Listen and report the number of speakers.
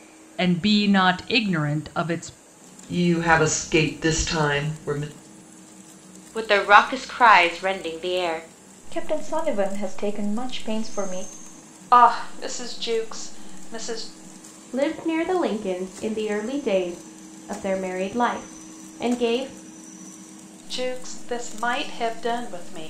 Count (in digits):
6